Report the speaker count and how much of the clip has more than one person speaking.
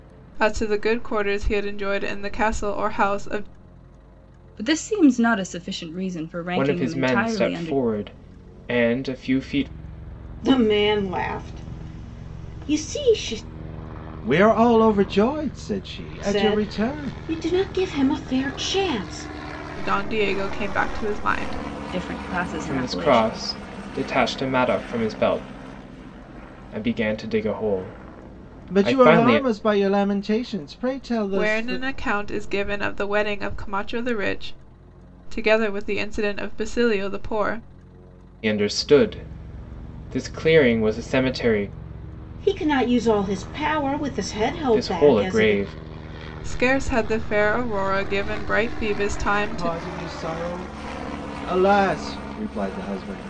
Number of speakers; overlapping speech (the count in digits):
5, about 11%